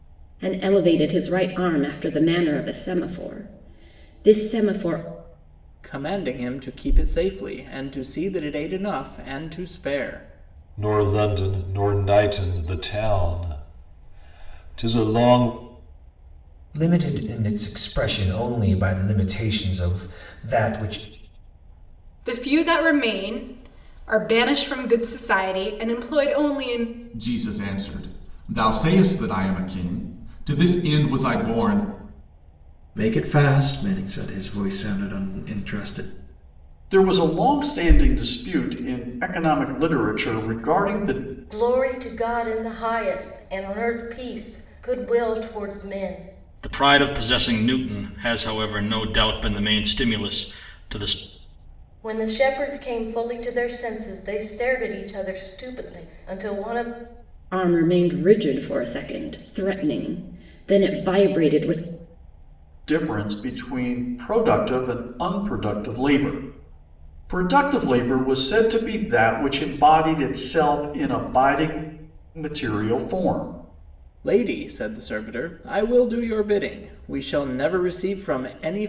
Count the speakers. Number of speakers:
10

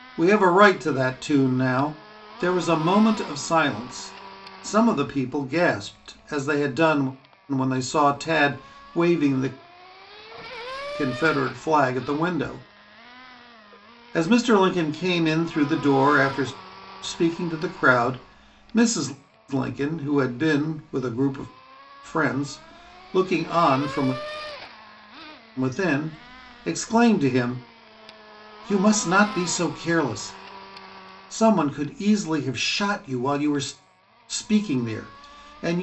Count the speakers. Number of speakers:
1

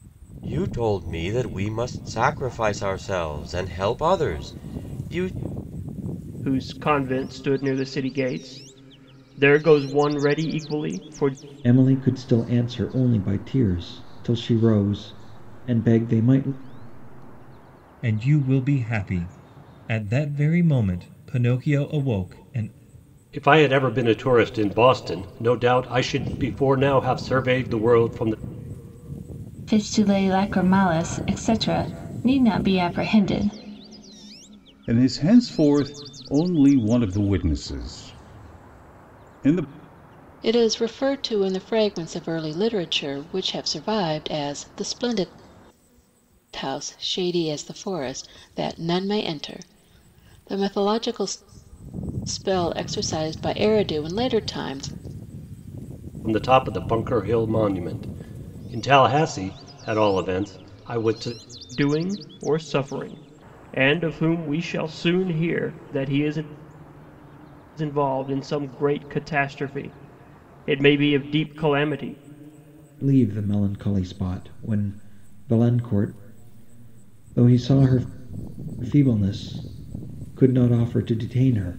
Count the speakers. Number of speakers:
8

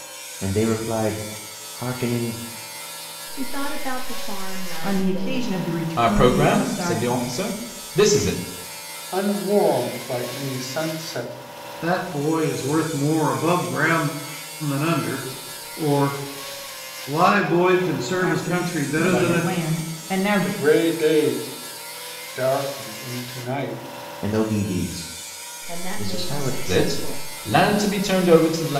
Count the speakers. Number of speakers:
6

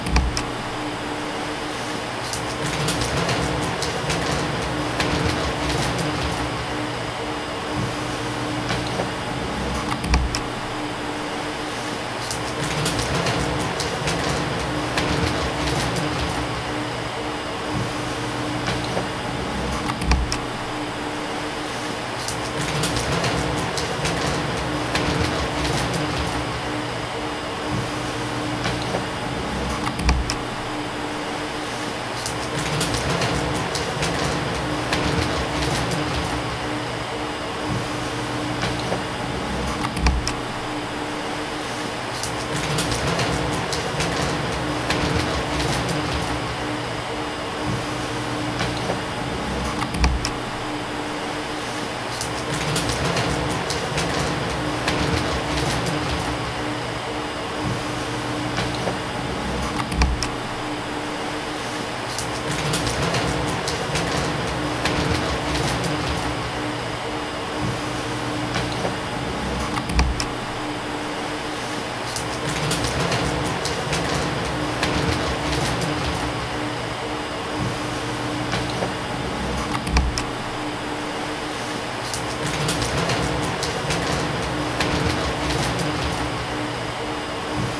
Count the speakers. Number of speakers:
0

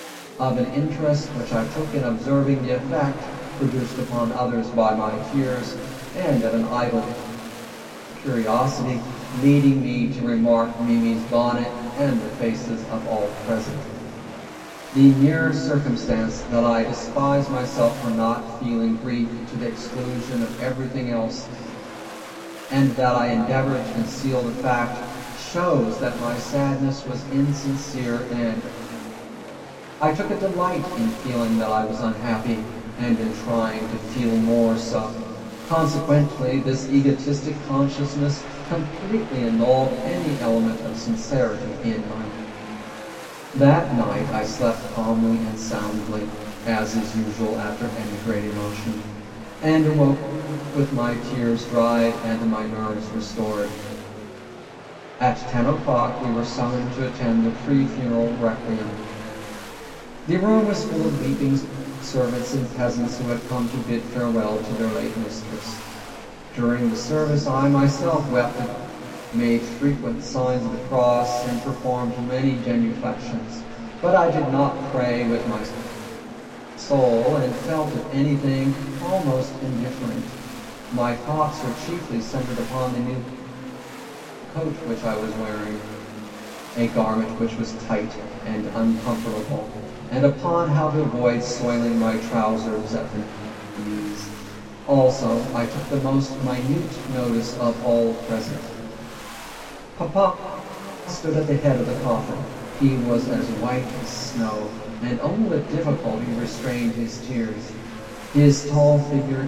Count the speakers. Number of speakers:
1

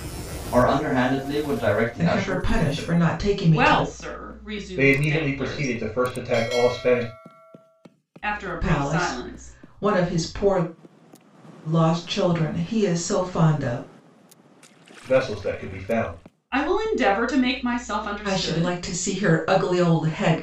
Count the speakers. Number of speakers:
4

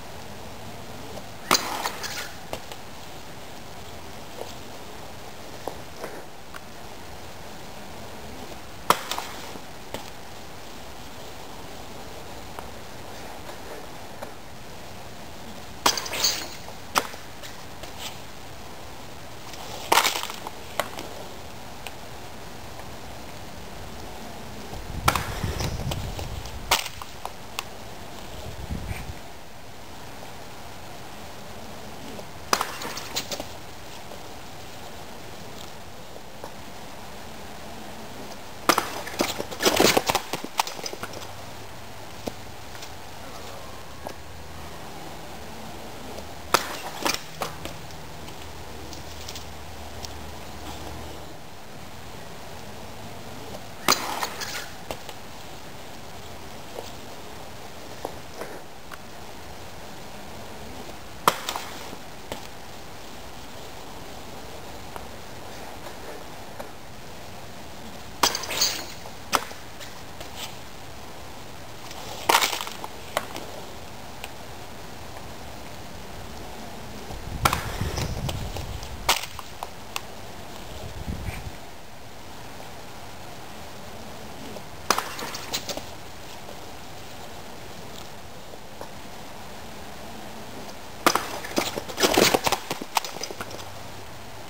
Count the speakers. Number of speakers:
0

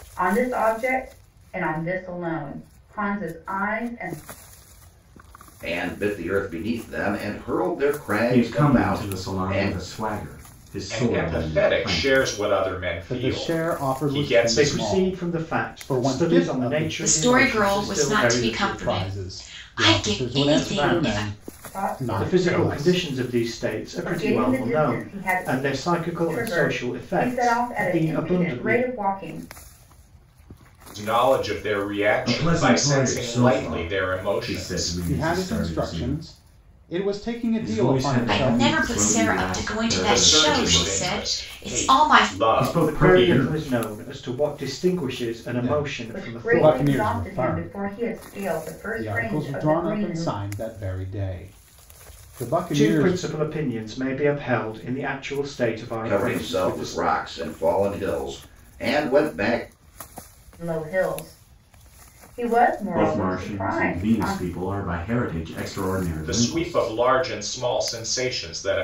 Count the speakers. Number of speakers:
7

